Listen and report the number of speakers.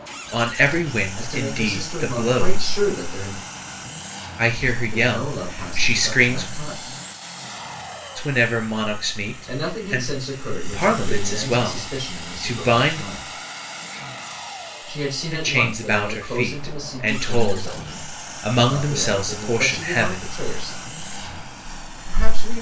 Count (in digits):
2